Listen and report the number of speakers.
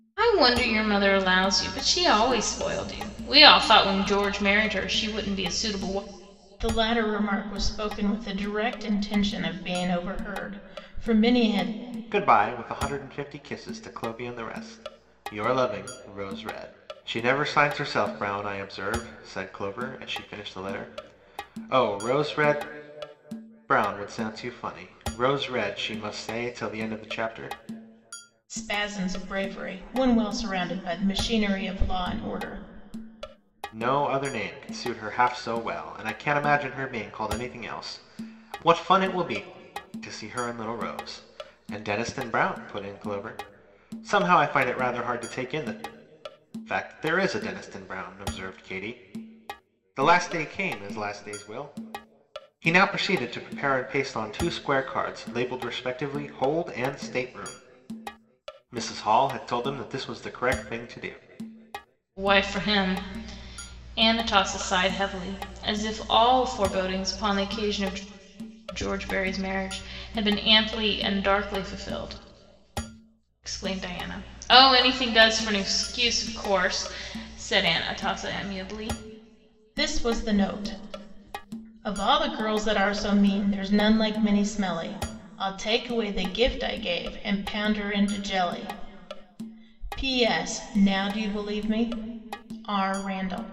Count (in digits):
3